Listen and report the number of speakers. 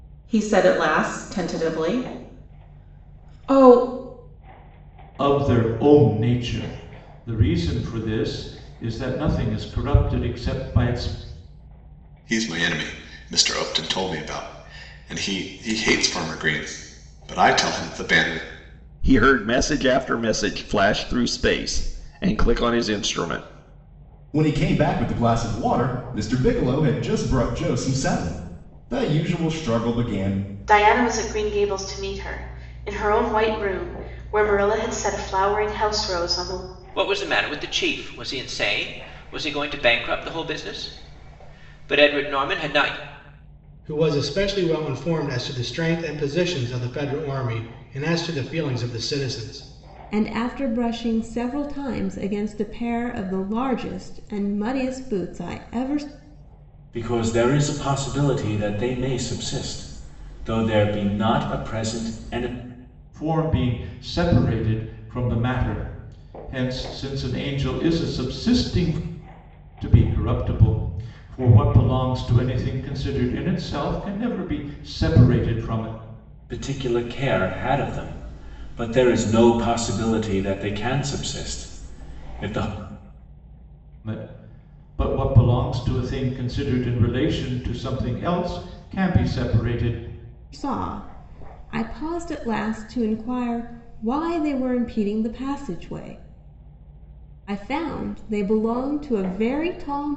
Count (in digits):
10